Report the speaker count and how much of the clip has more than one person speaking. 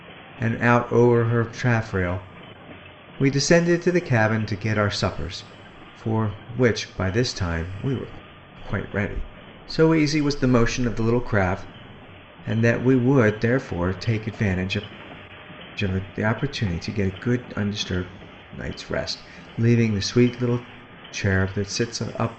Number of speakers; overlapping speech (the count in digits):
1, no overlap